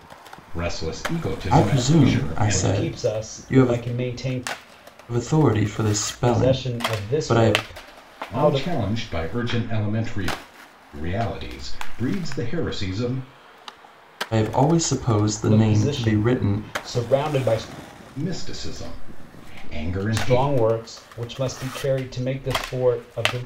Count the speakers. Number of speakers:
three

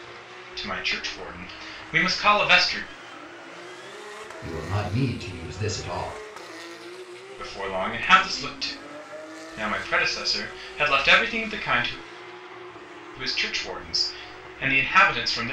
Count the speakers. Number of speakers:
two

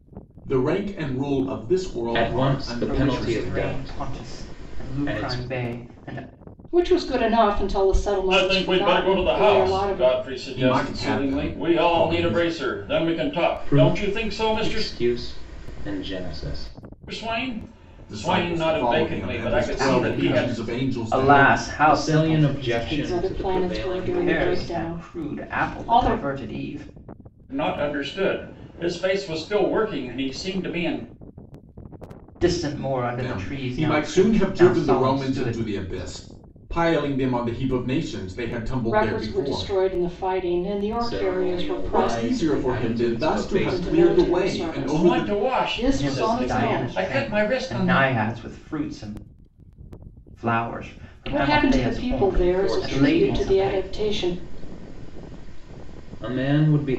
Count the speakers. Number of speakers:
five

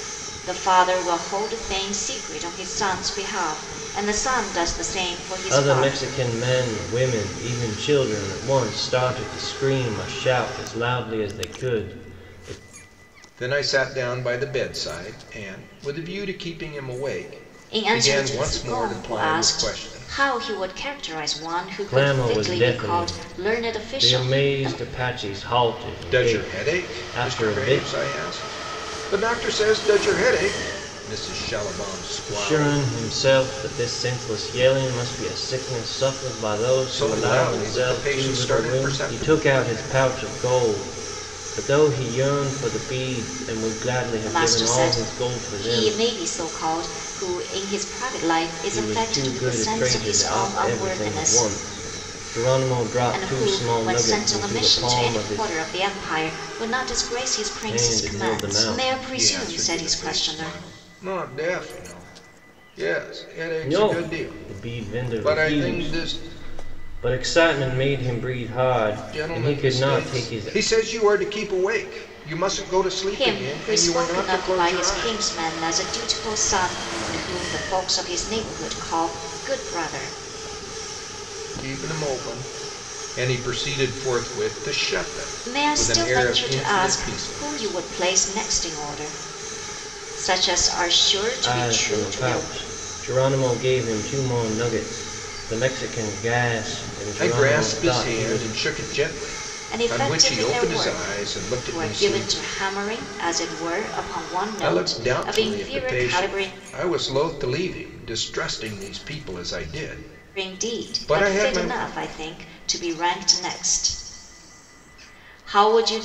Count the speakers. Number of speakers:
three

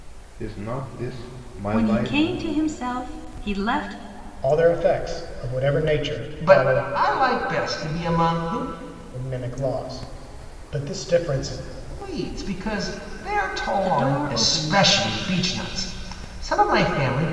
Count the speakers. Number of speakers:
four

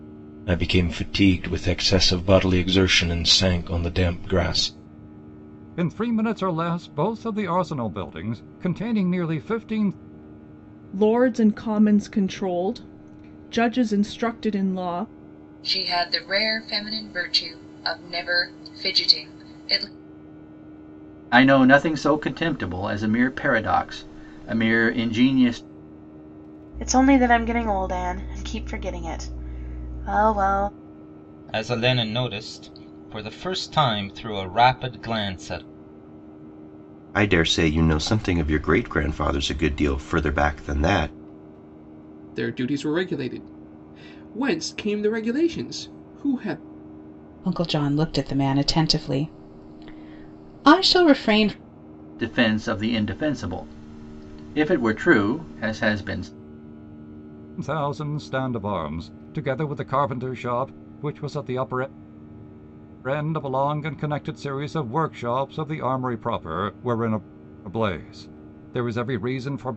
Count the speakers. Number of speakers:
ten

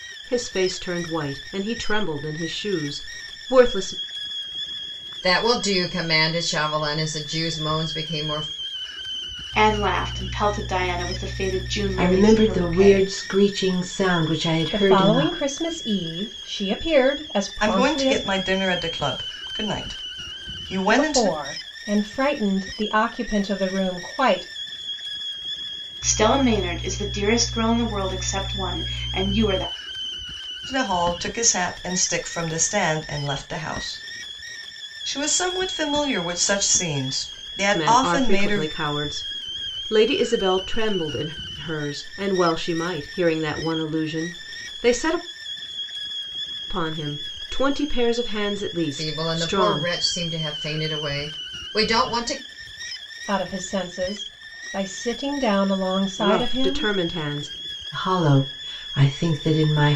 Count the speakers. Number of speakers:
six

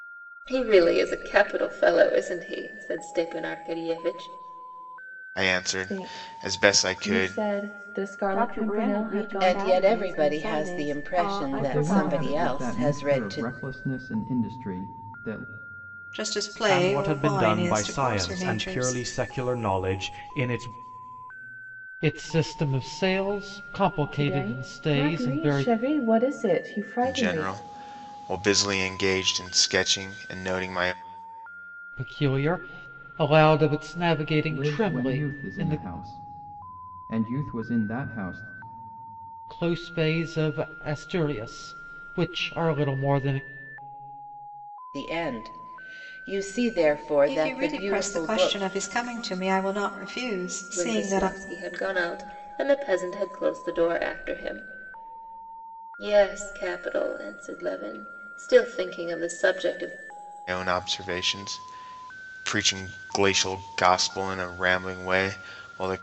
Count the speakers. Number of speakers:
nine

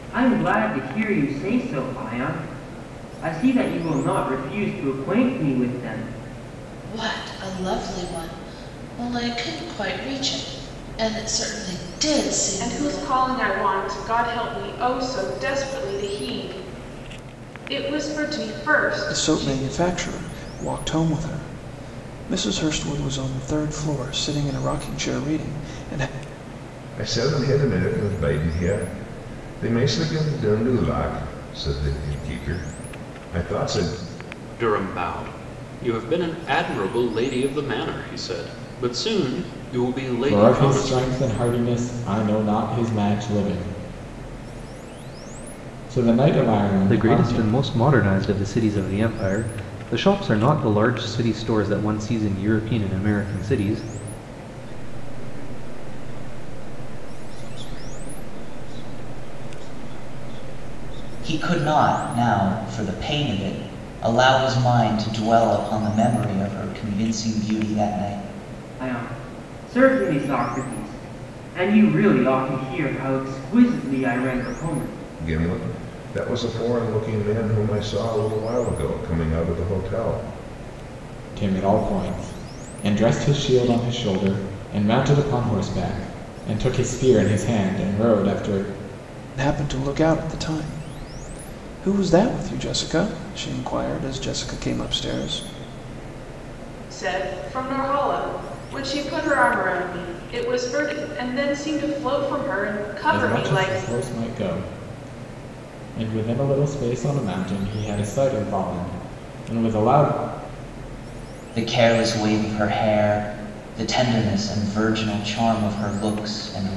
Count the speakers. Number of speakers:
ten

